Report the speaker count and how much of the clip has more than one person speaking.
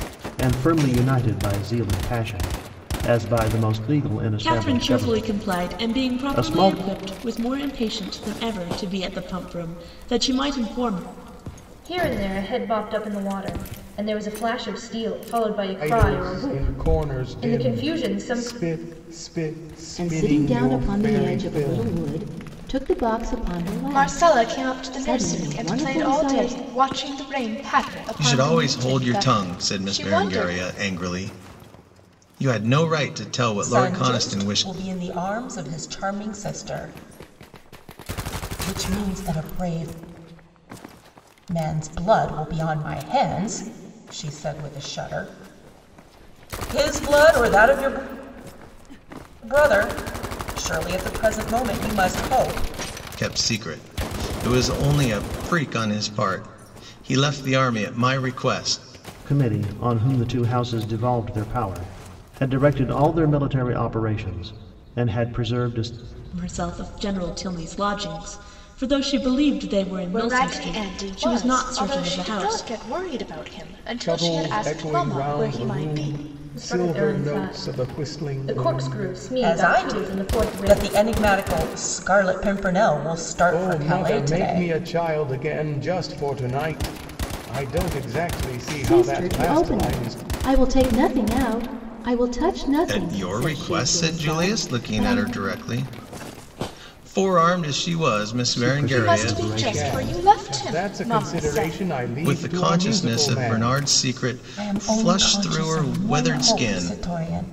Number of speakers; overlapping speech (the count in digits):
8, about 32%